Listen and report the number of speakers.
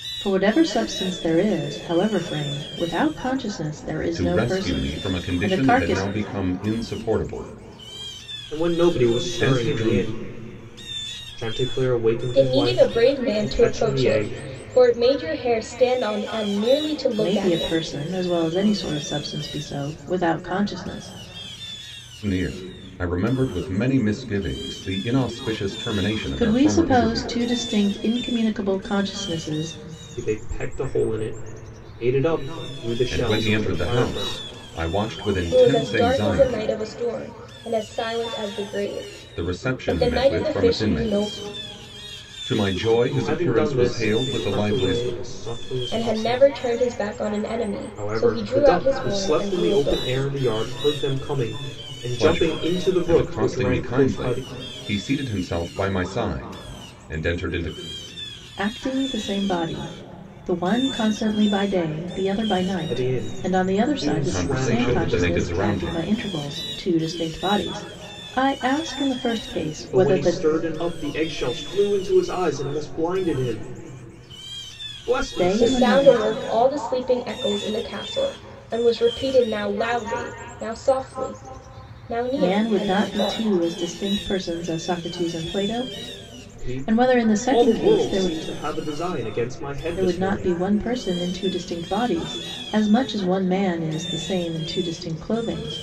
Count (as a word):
four